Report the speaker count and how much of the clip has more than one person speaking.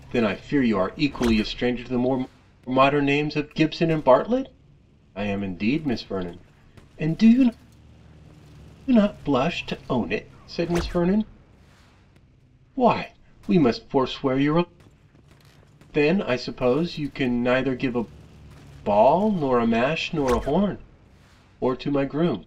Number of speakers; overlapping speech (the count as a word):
one, no overlap